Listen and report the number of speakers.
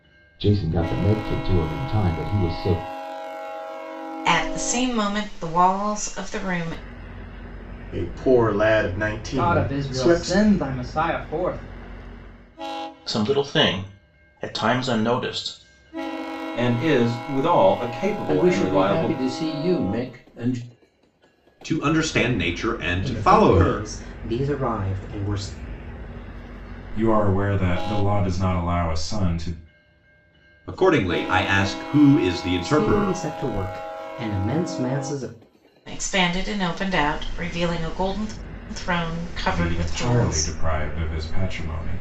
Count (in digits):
10